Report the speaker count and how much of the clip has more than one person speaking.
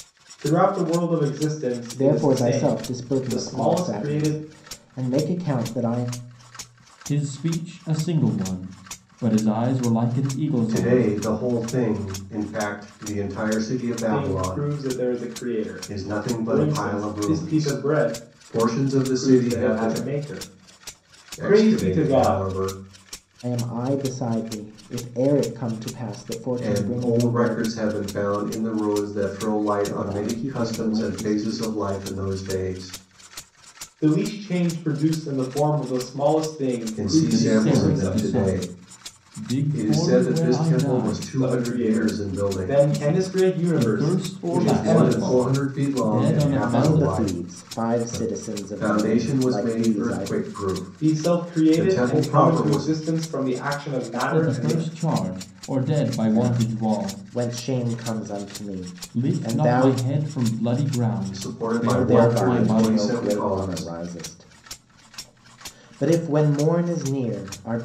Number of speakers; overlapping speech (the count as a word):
four, about 44%